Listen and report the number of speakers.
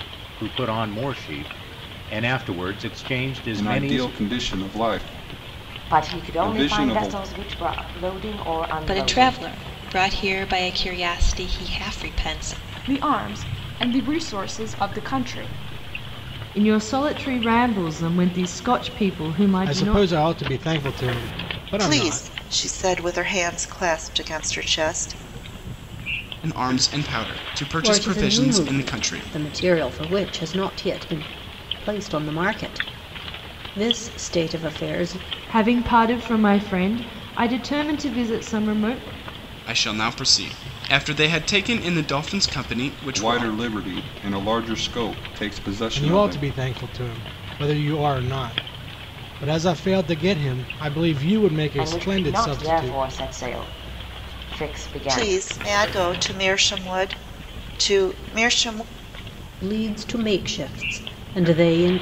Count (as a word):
ten